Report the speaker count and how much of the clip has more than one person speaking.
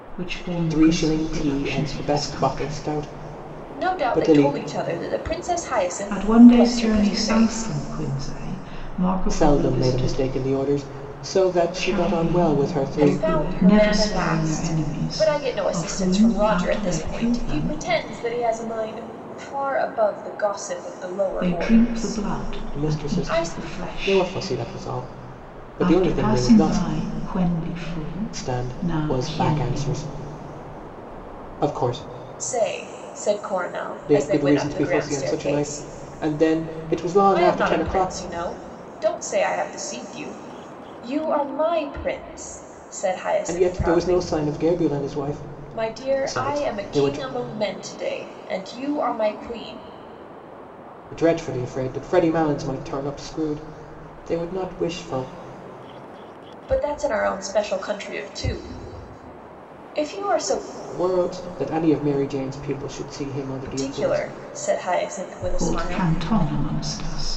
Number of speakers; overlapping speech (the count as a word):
three, about 35%